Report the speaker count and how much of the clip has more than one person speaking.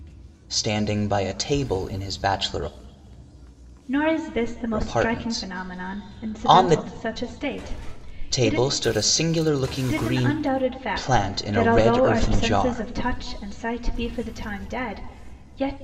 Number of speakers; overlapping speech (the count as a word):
two, about 31%